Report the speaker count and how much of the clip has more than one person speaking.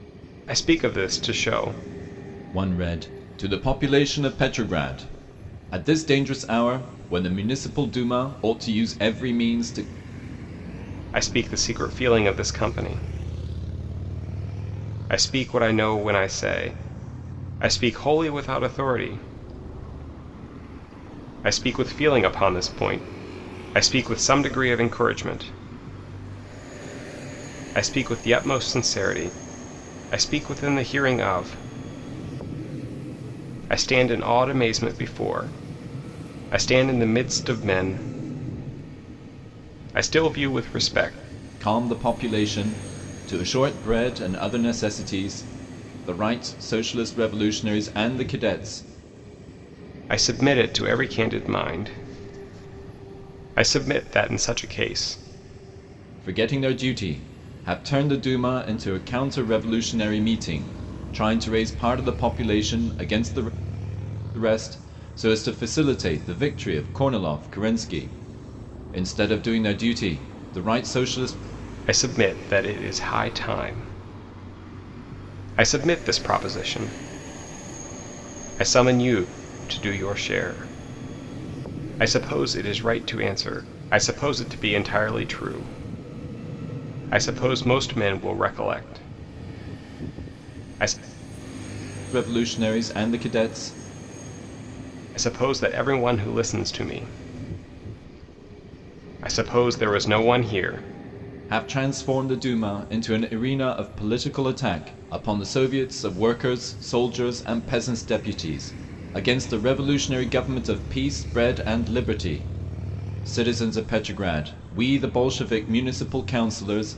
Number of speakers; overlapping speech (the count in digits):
2, no overlap